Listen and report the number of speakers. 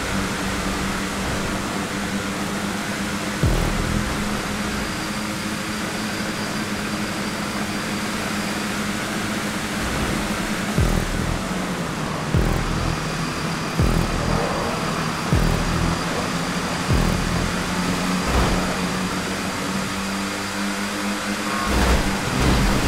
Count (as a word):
zero